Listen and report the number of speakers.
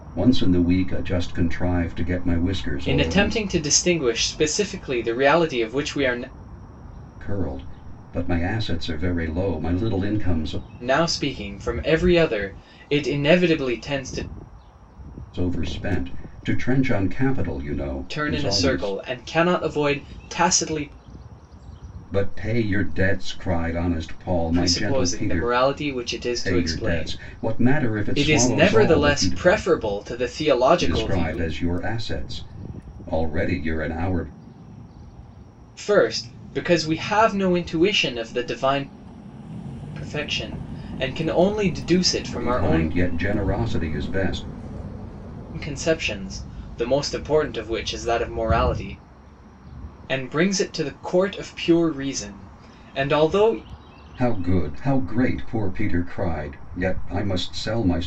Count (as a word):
two